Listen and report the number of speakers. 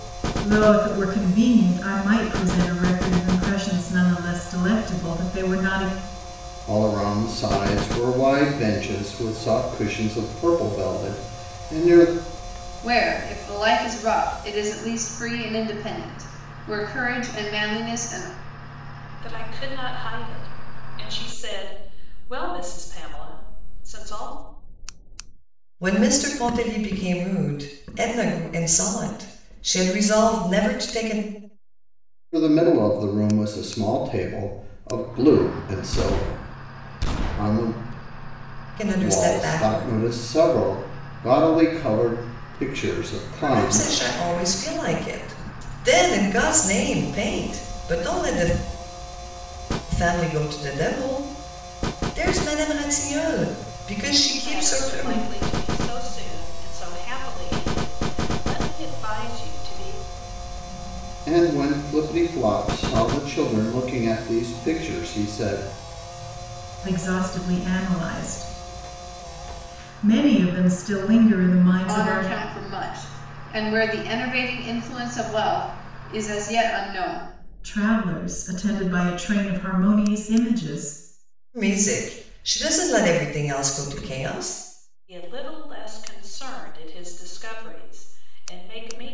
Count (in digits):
5